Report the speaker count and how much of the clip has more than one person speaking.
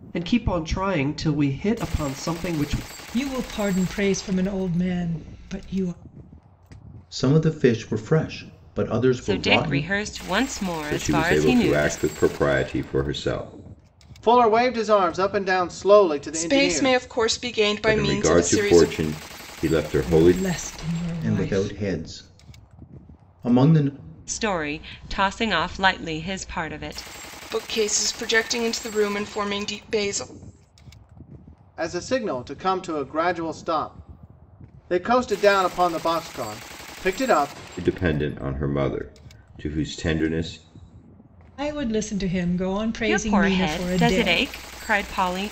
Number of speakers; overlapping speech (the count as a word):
seven, about 13%